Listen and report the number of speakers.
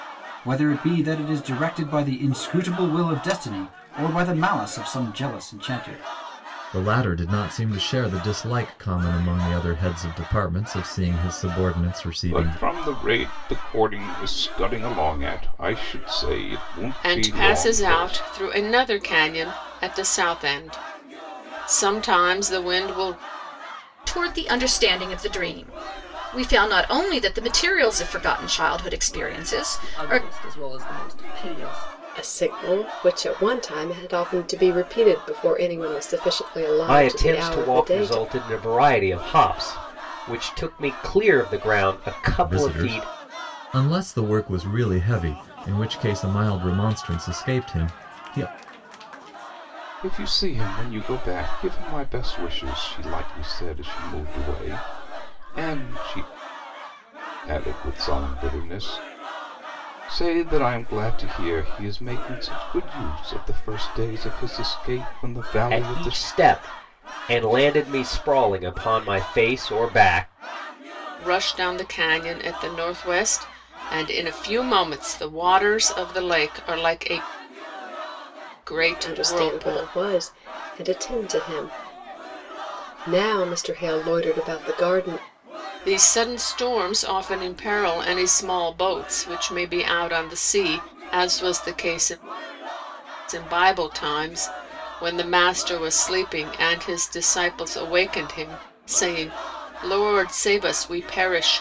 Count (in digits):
8